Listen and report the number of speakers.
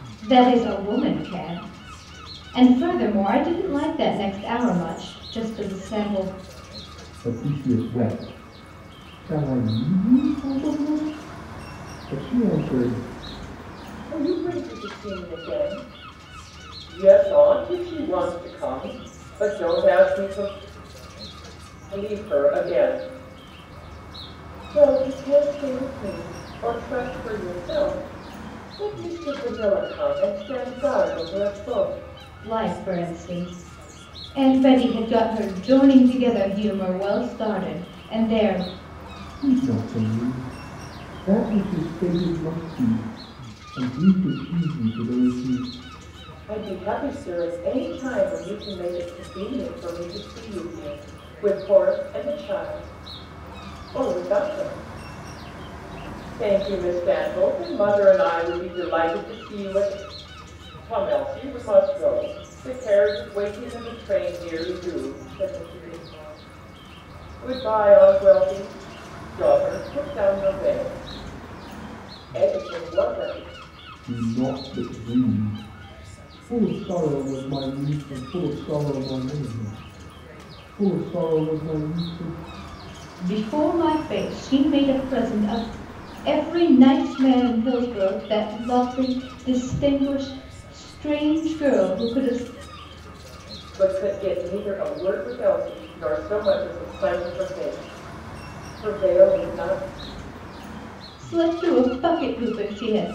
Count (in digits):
3